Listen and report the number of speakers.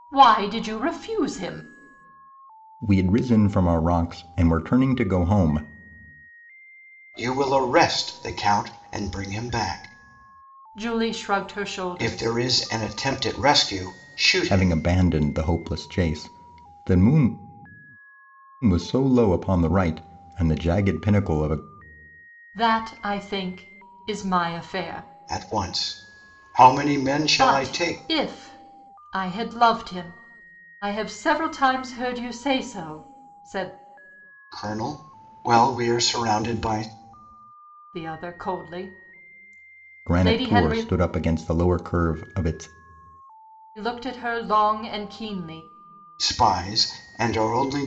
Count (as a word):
three